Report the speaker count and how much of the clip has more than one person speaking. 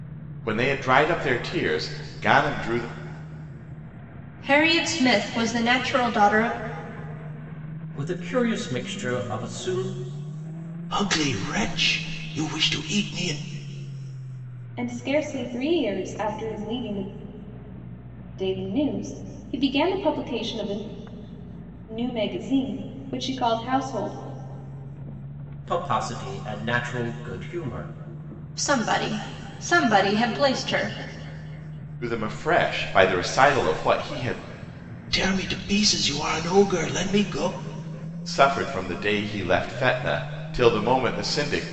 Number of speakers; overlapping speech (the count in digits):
5, no overlap